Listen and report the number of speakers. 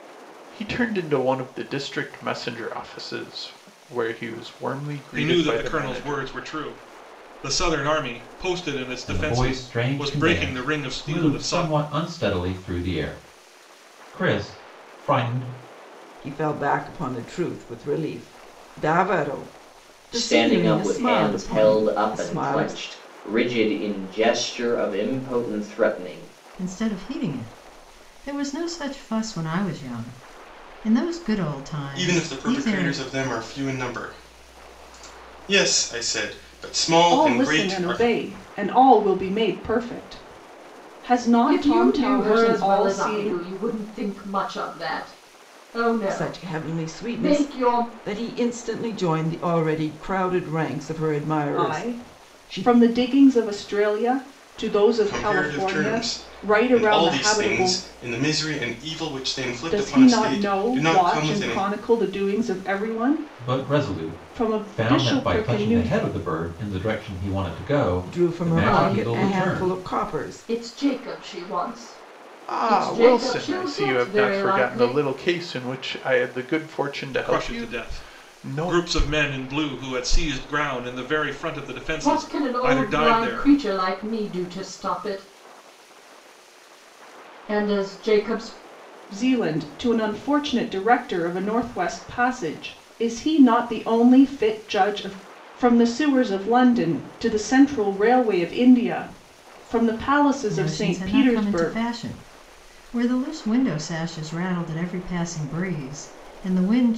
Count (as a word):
nine